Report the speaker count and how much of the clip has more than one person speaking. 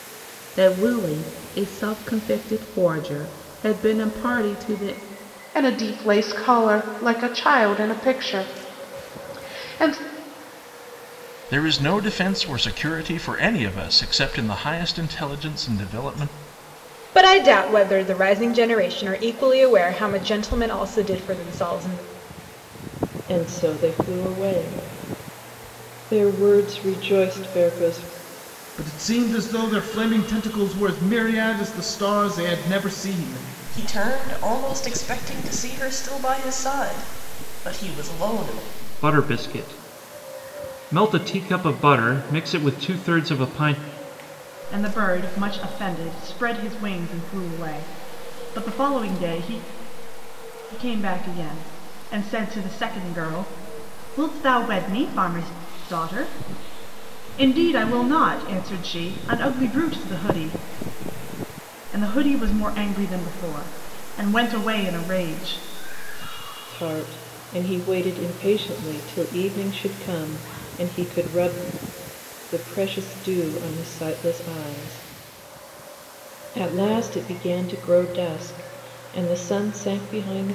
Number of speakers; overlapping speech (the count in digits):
9, no overlap